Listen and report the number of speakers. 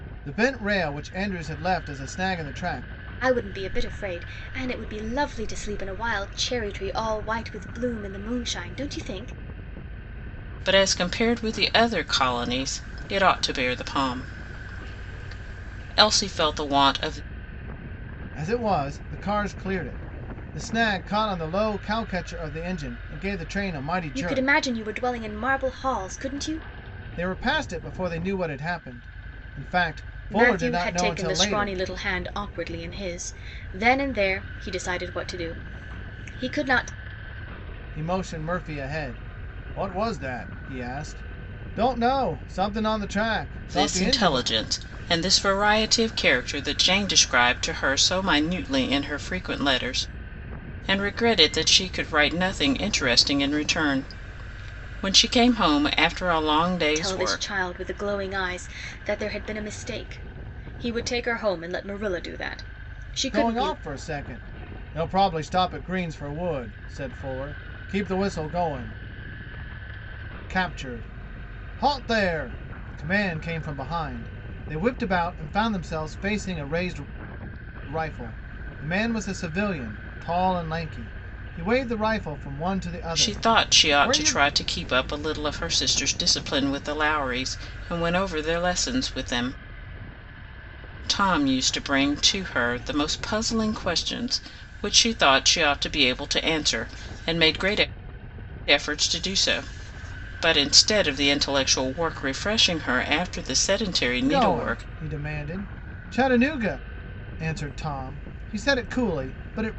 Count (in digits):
3